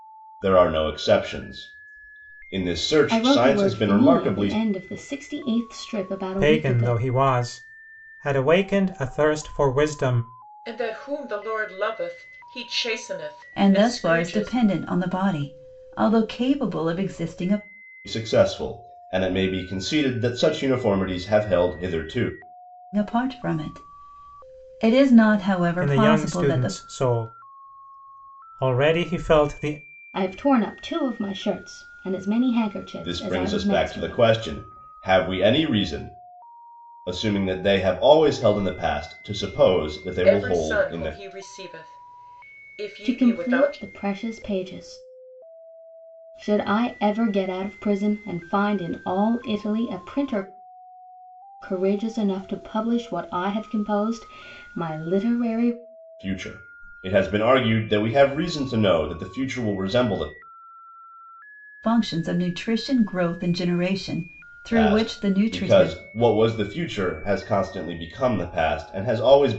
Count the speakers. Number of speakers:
5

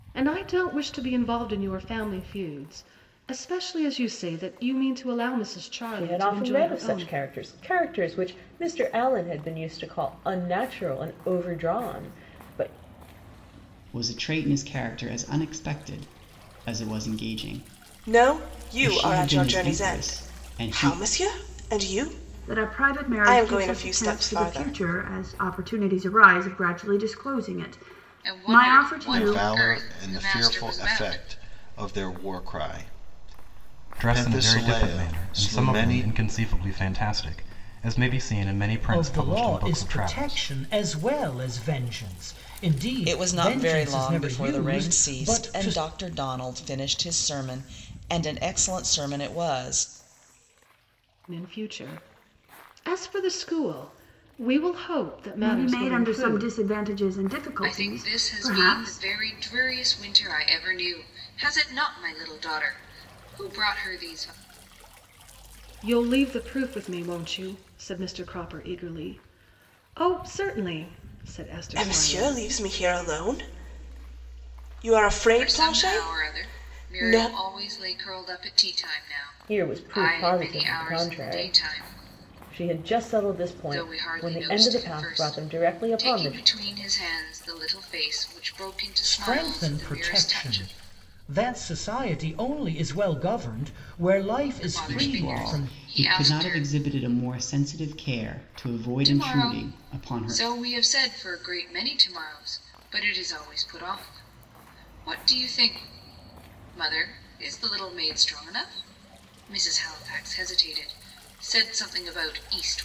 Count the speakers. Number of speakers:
10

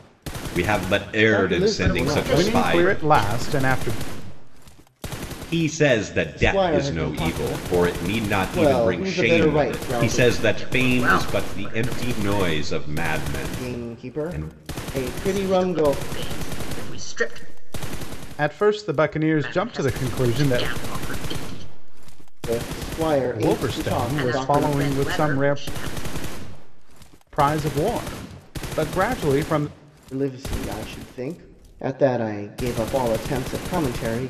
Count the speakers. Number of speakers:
4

